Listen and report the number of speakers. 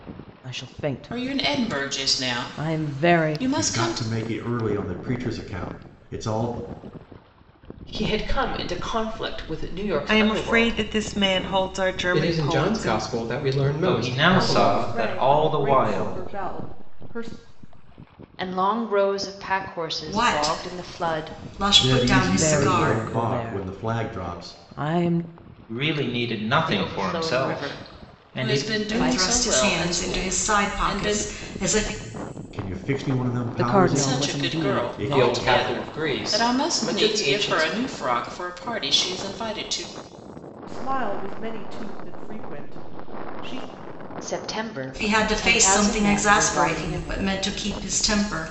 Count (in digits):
10